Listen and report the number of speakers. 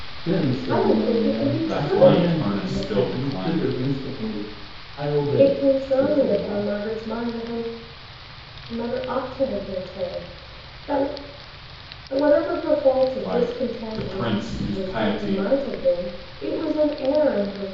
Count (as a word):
three